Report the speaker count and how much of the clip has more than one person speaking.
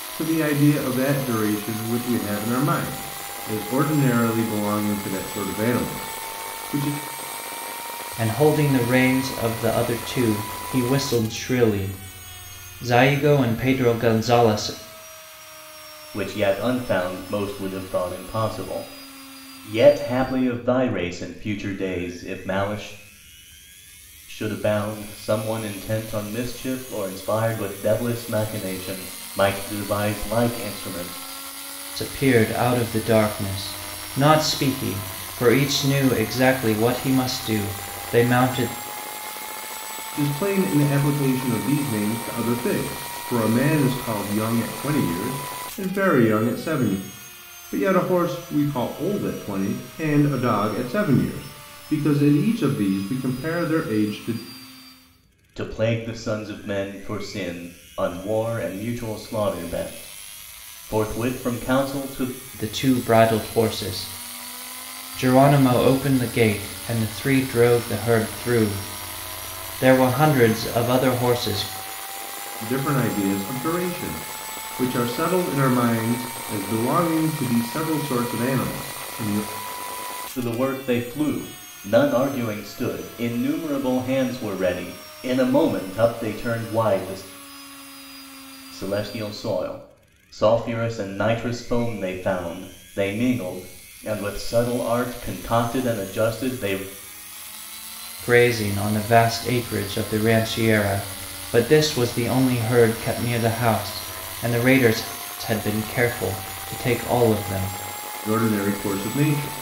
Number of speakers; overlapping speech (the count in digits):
3, no overlap